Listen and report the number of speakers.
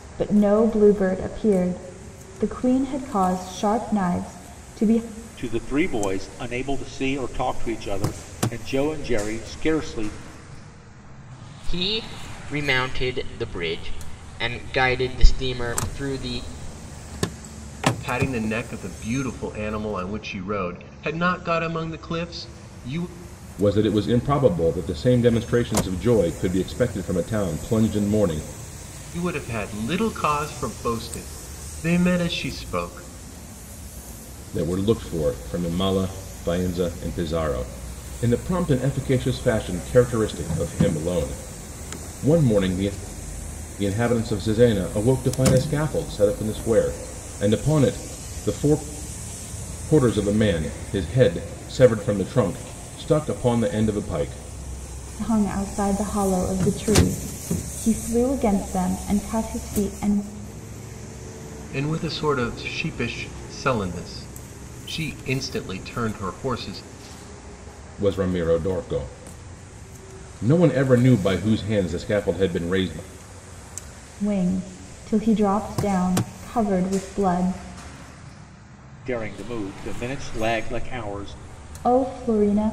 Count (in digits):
5